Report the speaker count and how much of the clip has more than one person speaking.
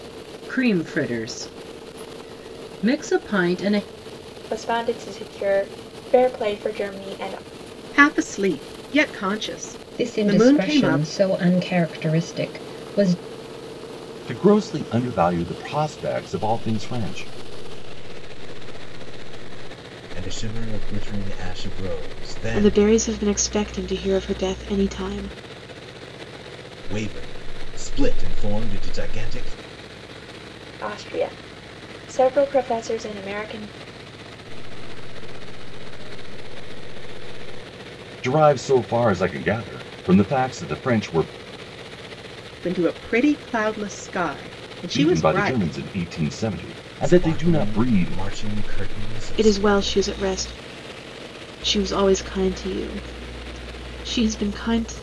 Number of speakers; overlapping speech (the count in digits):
8, about 9%